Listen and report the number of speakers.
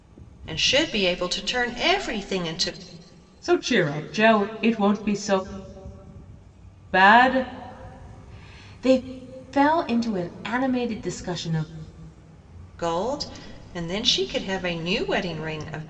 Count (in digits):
2